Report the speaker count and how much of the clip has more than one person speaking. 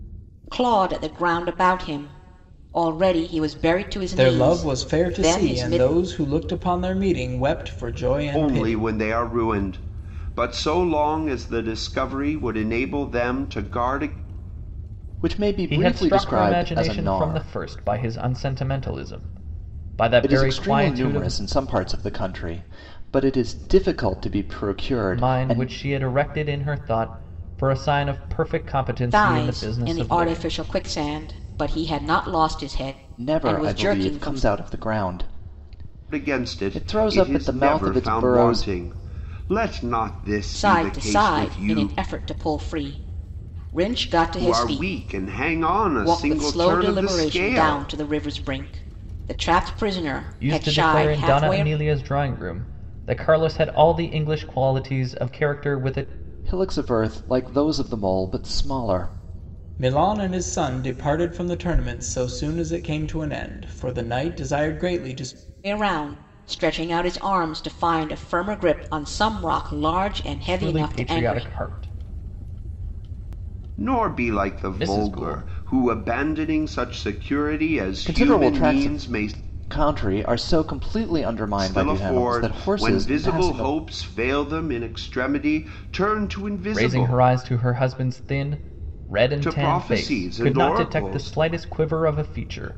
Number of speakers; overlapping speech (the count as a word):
five, about 27%